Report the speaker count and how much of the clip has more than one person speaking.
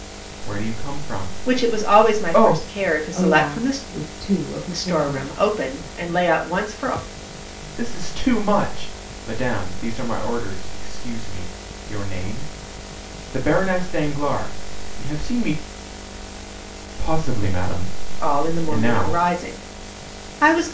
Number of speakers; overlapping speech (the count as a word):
three, about 17%